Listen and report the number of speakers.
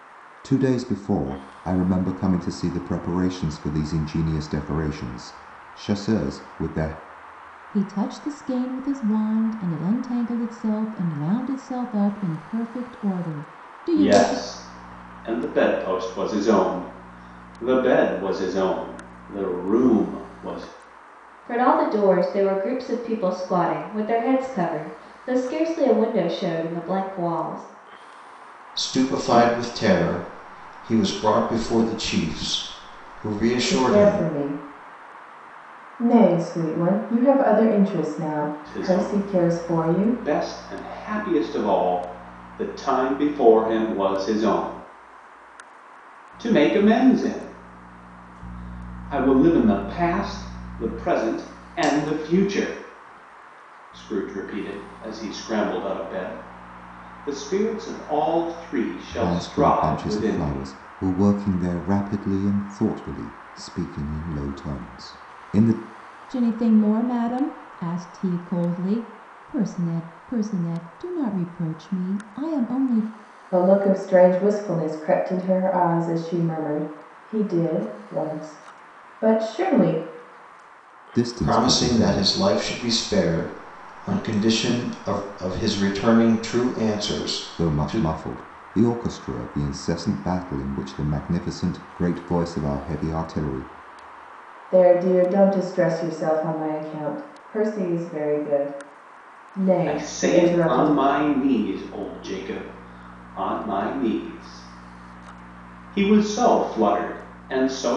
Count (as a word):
six